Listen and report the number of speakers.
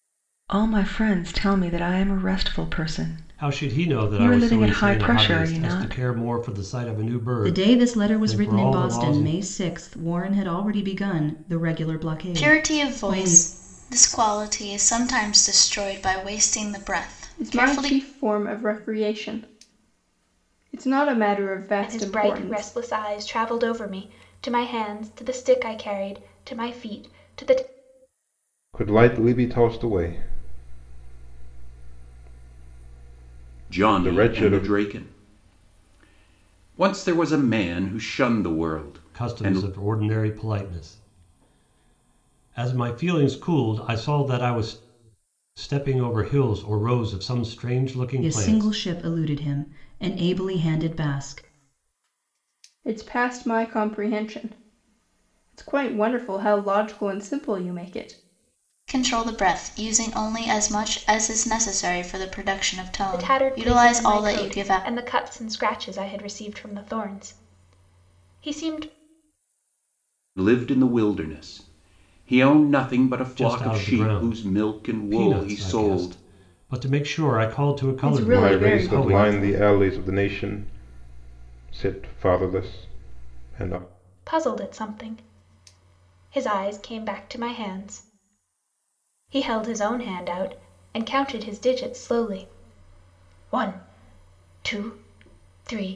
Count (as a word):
eight